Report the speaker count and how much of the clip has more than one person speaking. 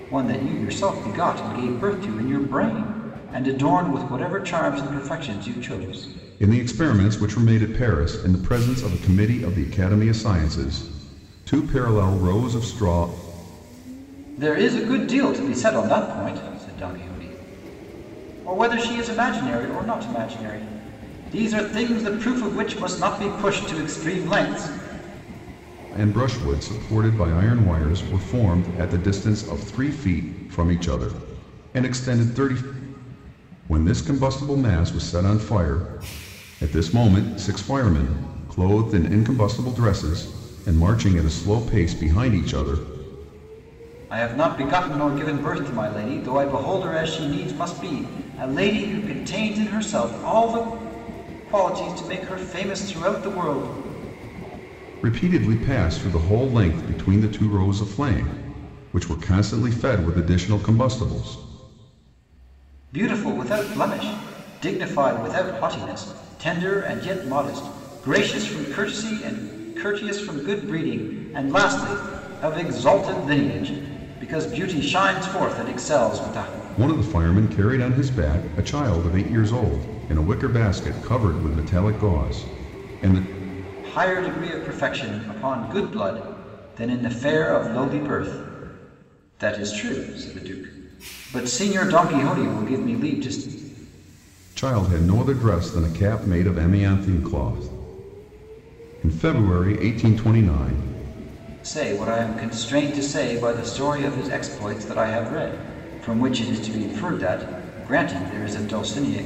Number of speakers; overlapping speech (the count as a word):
two, no overlap